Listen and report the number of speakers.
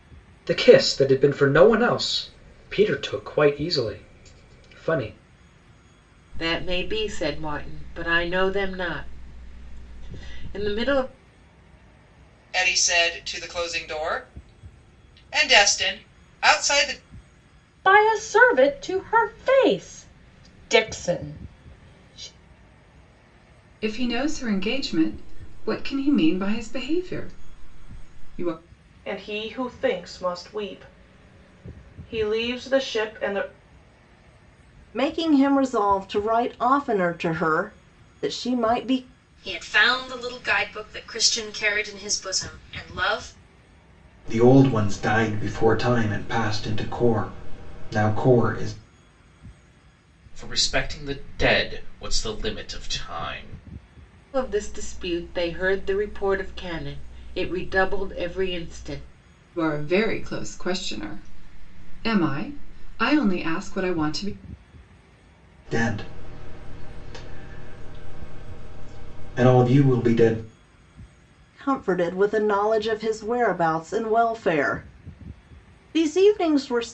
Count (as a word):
ten